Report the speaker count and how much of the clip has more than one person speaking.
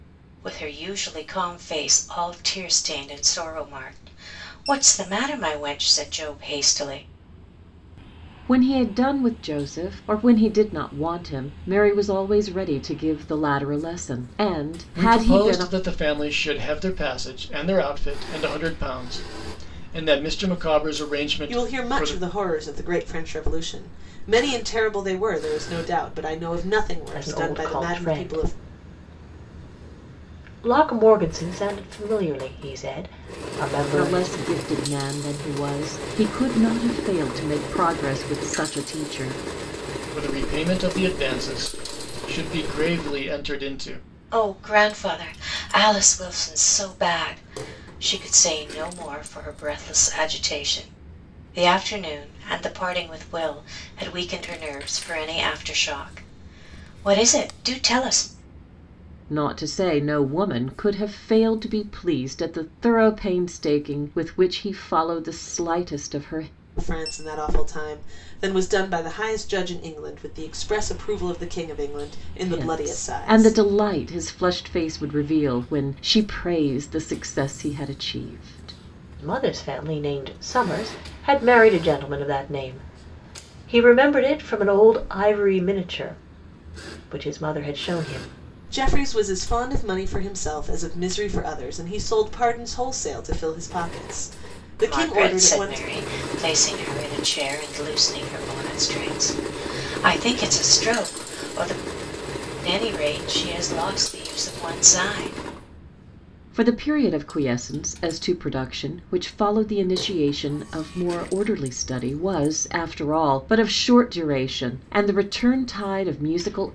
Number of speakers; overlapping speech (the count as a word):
five, about 5%